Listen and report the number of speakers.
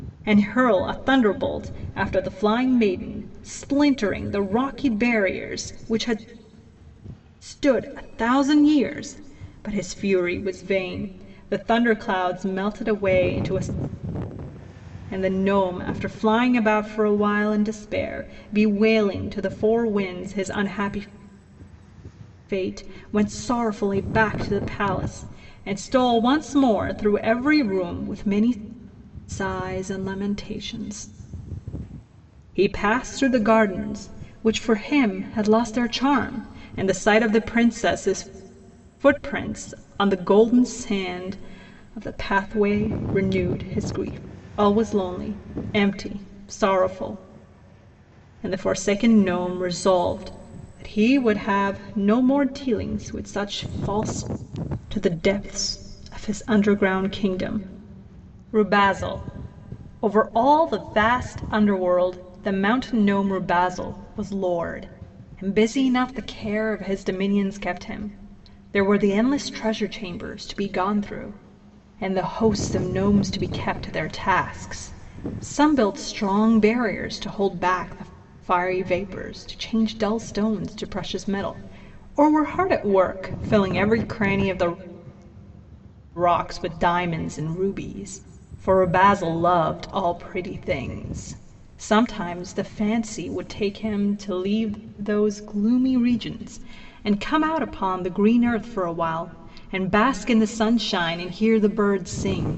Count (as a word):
one